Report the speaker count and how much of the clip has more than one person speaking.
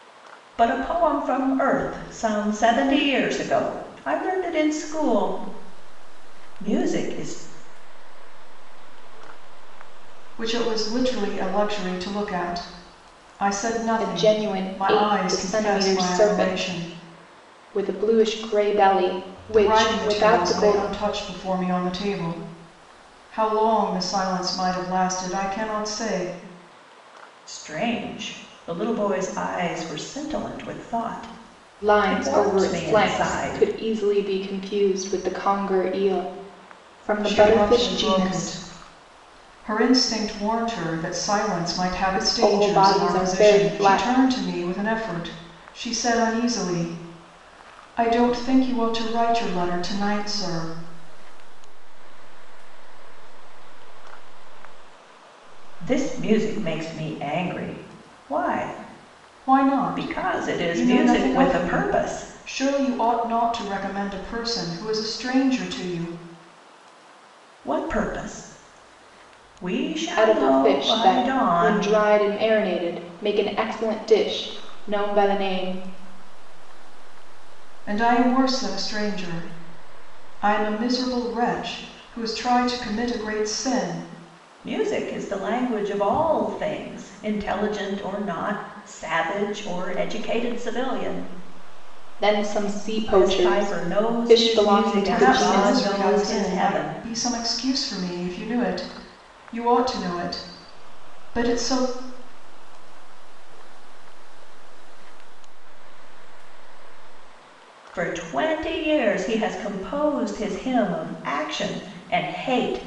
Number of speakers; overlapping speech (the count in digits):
4, about 30%